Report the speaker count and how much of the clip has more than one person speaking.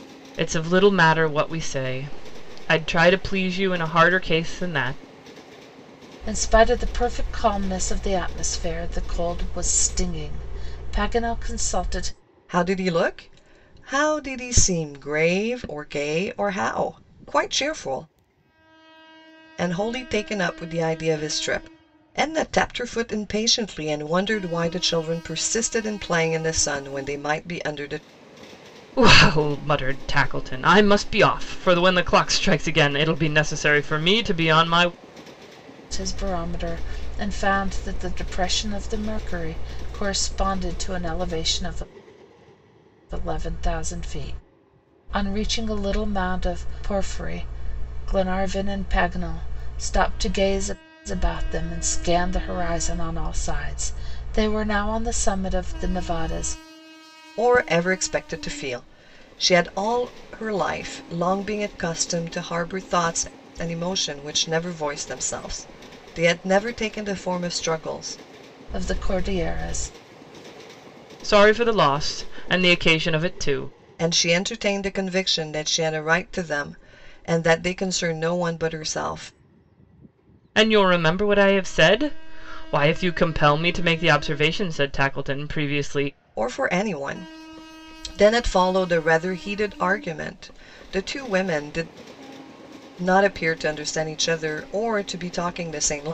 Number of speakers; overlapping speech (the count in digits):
3, no overlap